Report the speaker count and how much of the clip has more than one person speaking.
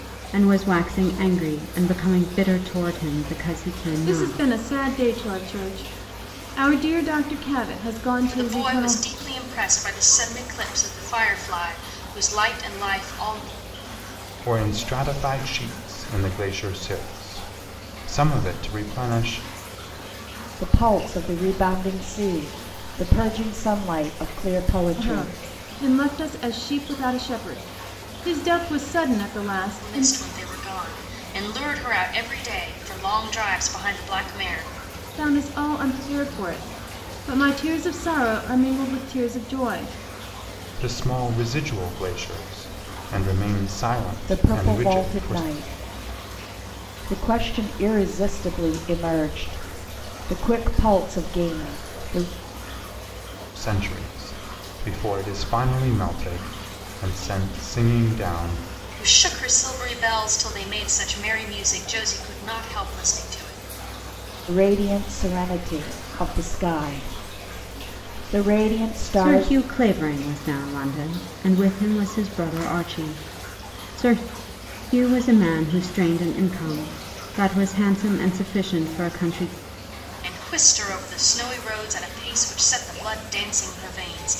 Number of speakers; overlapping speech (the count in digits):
5, about 4%